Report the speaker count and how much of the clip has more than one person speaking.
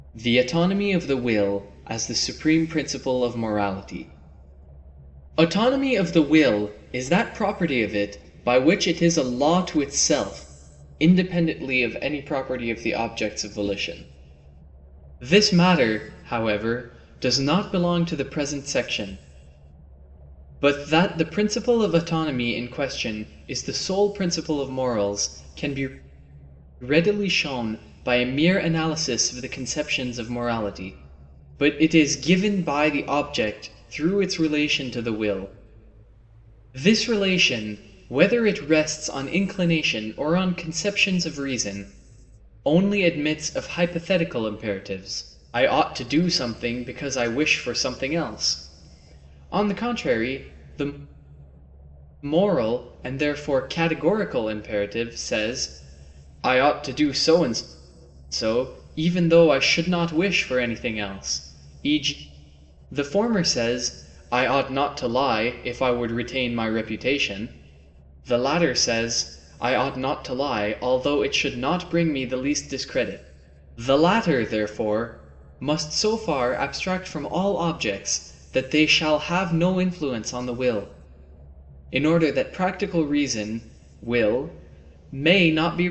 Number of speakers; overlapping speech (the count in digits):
1, no overlap